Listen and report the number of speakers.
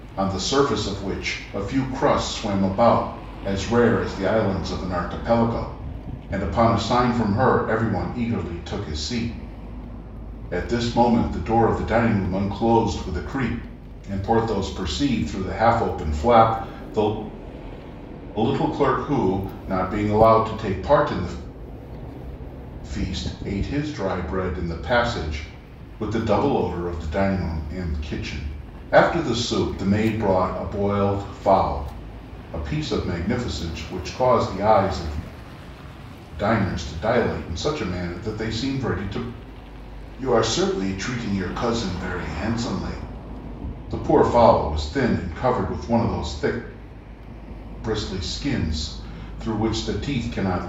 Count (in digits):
1